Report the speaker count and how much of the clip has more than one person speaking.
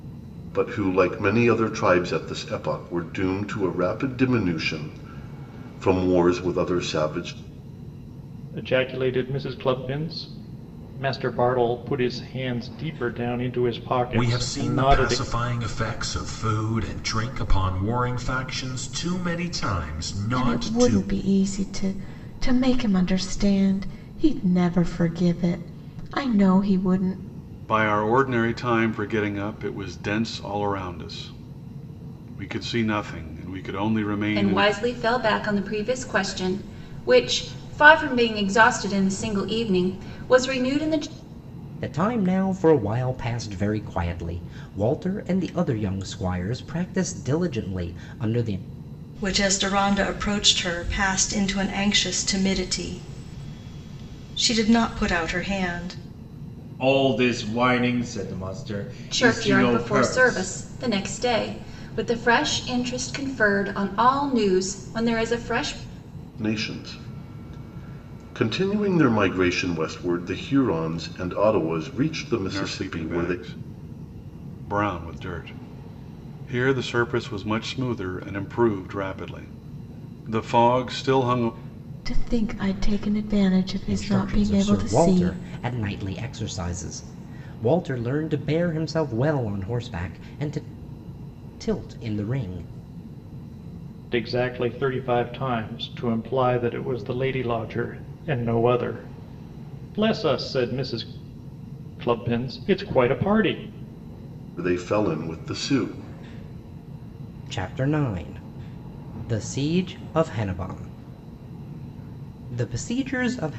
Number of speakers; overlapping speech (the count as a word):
nine, about 5%